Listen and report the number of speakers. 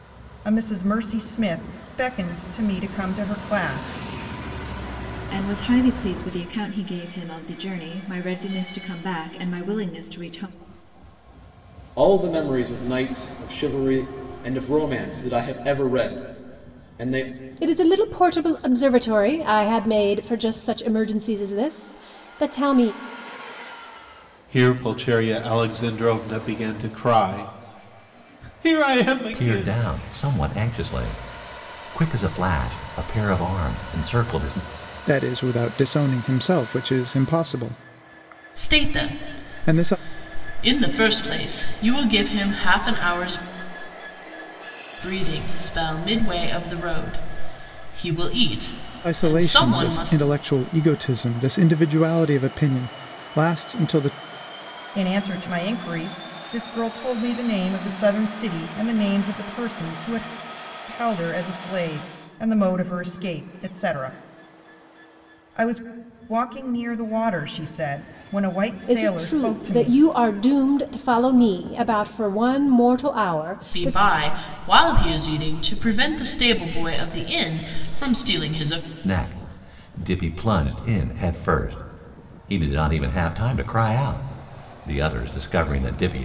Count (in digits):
8